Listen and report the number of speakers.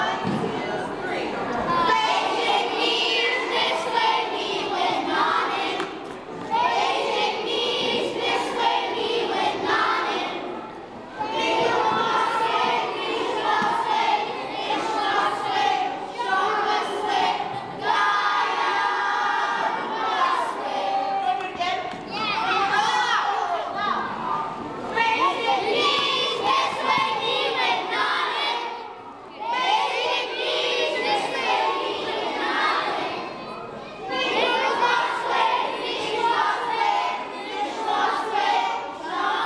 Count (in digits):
0